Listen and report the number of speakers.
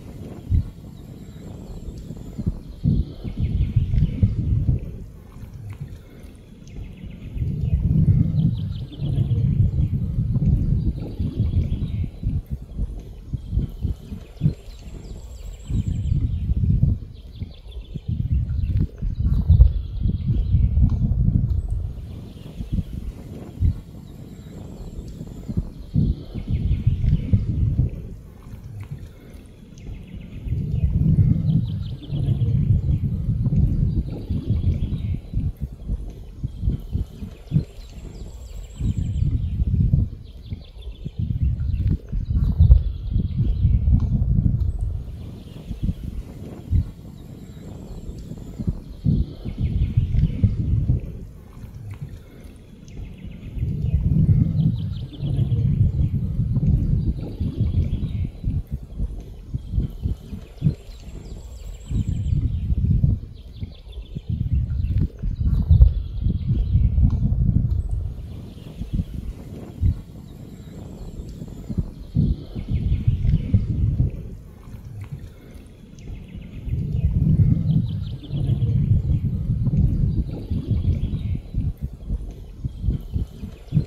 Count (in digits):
0